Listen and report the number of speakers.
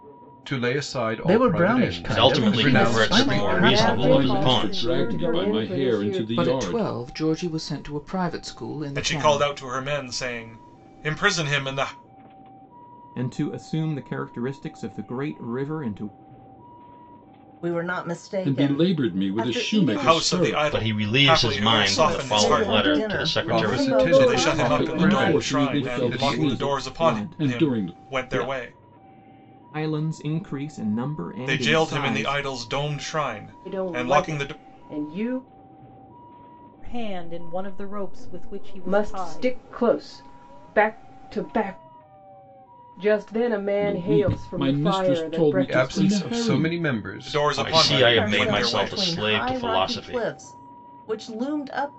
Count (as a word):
ten